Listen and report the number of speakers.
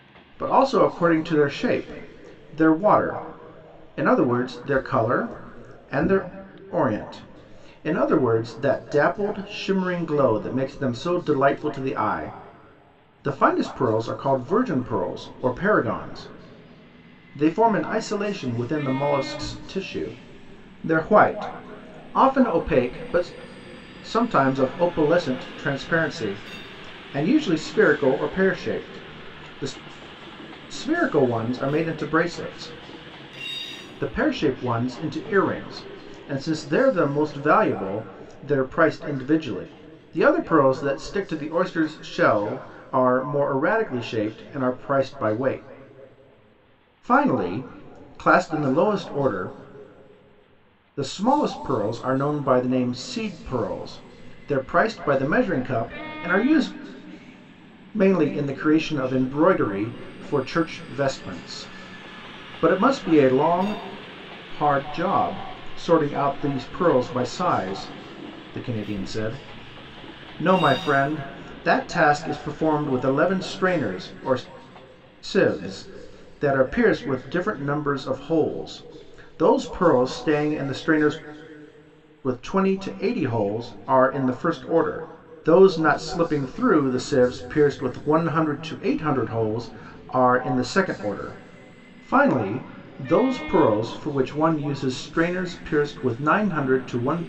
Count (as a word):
one